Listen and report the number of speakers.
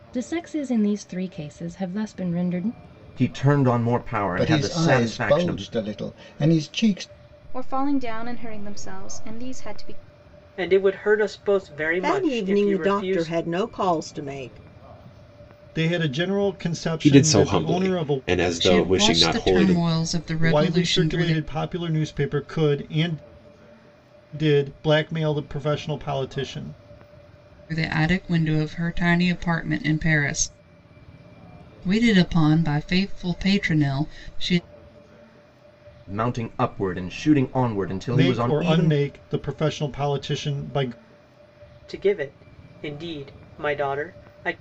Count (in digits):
9